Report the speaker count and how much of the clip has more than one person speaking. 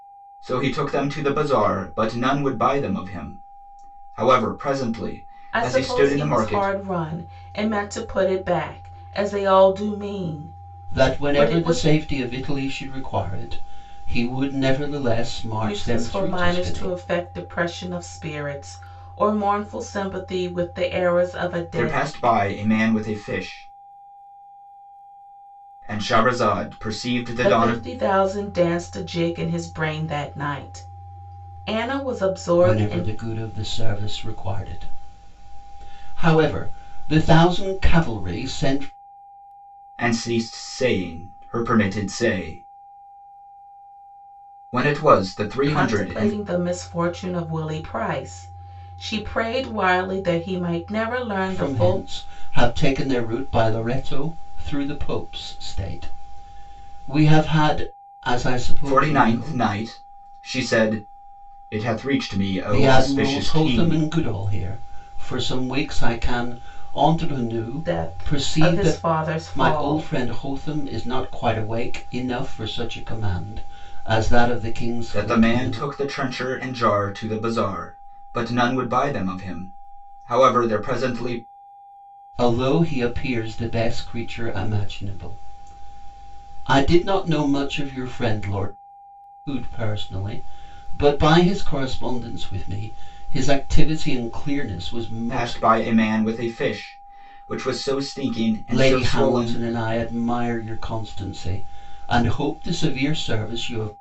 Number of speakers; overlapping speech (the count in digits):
3, about 12%